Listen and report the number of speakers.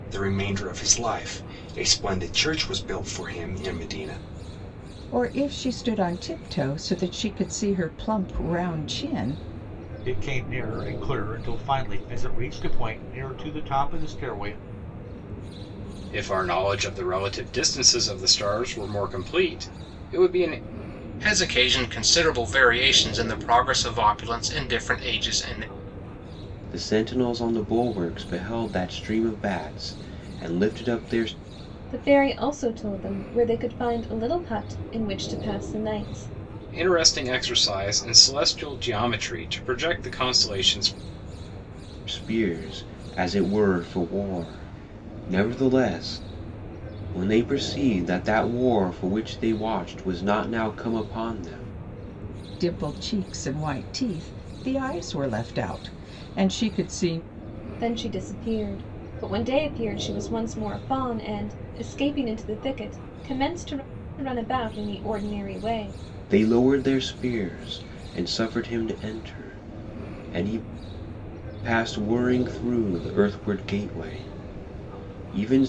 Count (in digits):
7